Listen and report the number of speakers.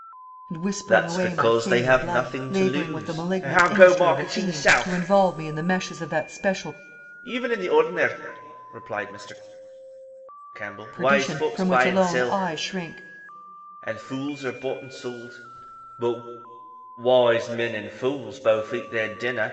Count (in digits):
2